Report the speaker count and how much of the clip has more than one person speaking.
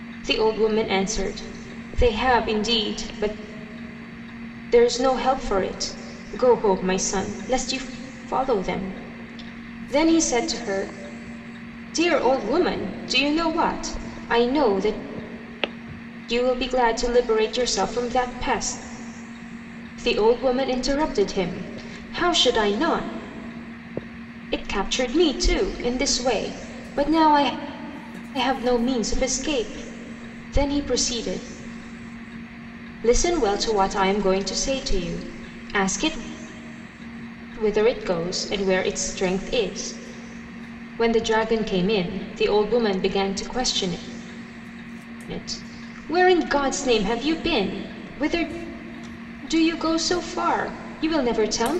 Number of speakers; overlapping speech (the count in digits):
1, no overlap